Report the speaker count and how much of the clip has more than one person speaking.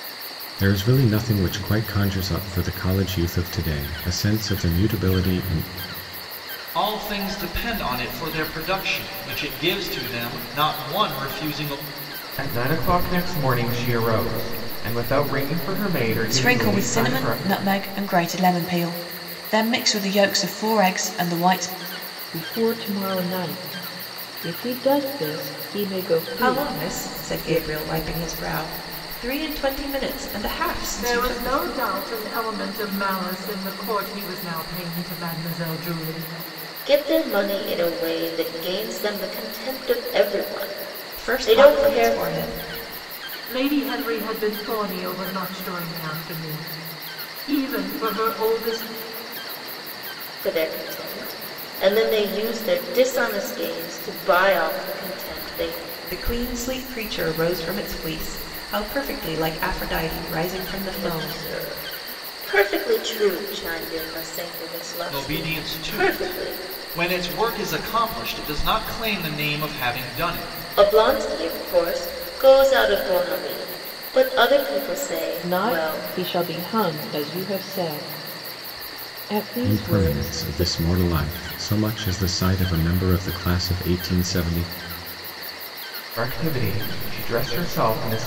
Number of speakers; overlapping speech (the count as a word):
eight, about 9%